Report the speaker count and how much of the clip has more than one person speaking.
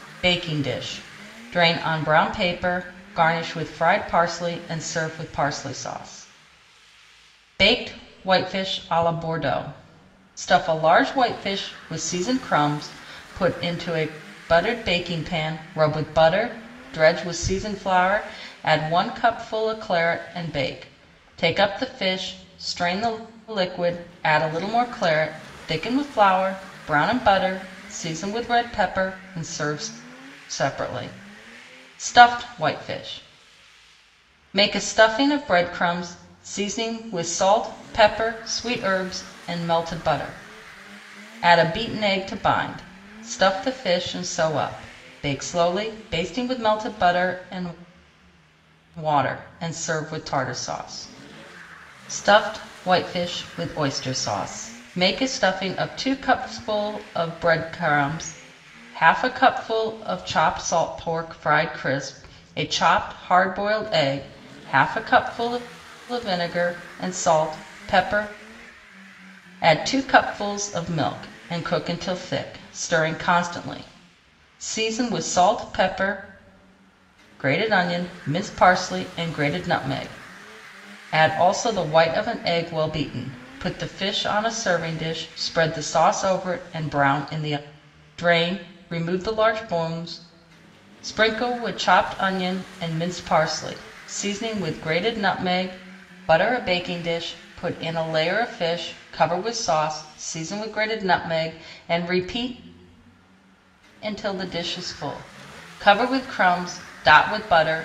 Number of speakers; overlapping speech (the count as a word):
one, no overlap